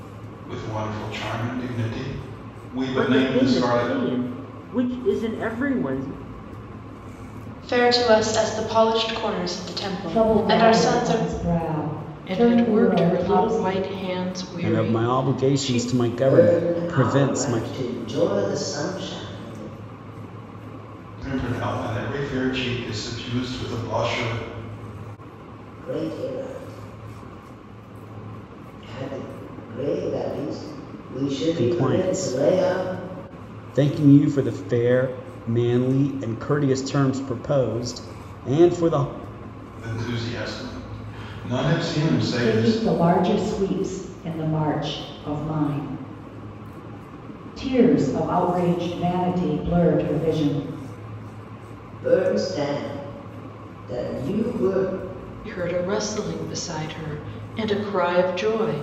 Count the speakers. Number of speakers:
seven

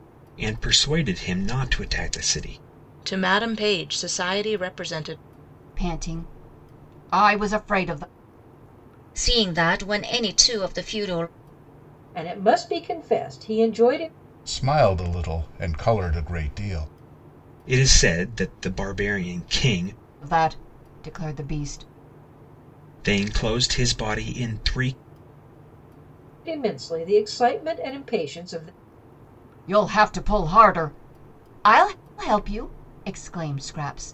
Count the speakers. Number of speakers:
six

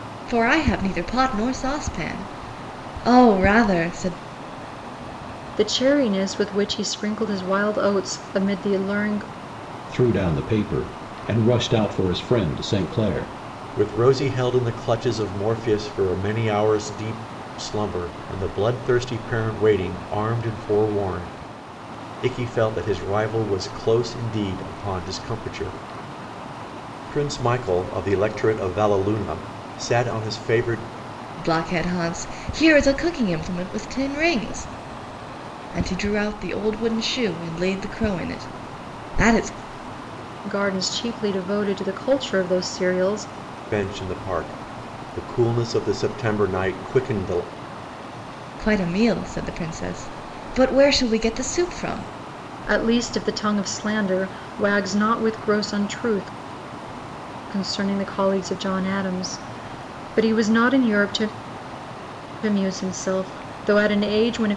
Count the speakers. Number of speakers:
four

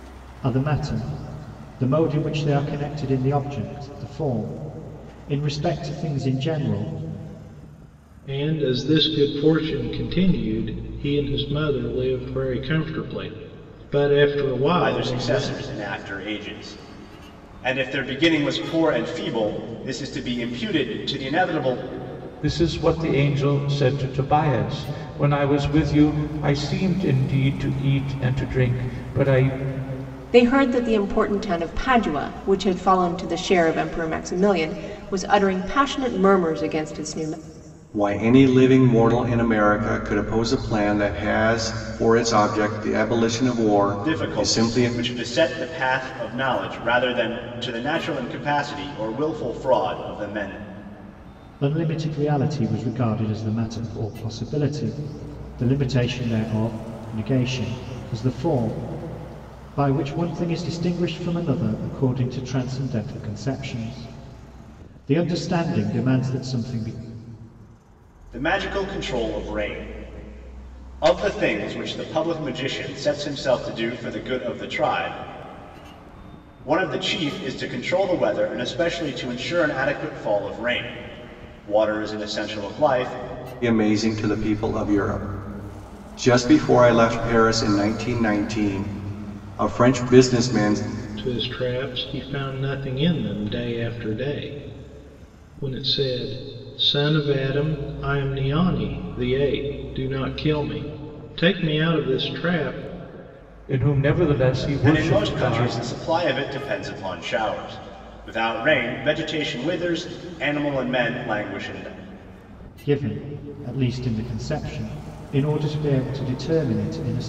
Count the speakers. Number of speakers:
six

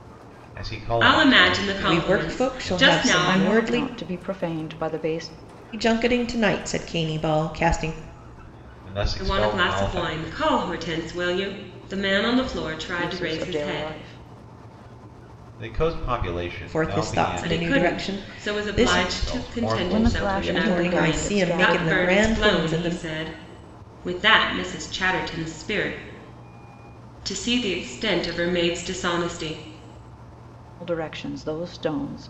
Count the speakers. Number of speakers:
four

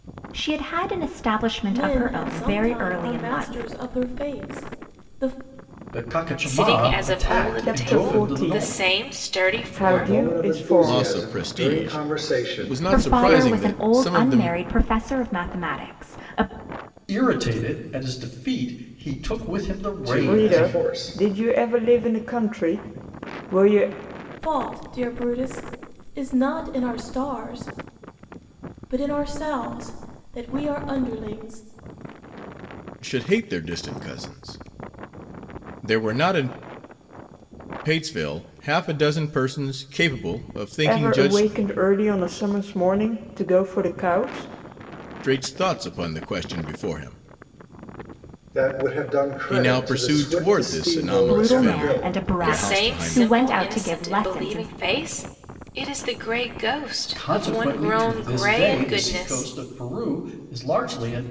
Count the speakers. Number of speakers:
seven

